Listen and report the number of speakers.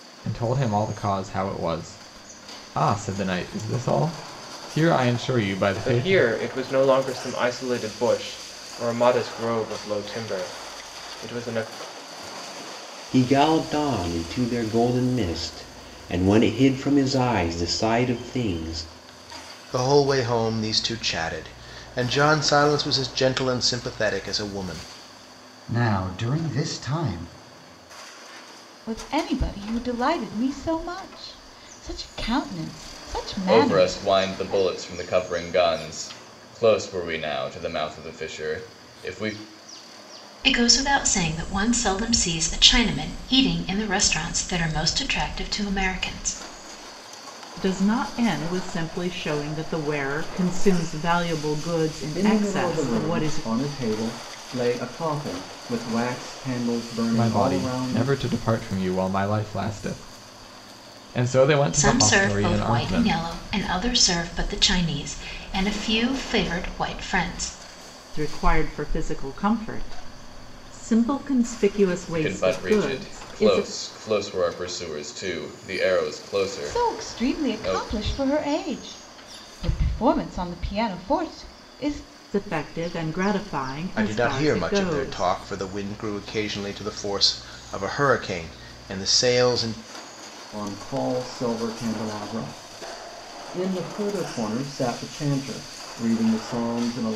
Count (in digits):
10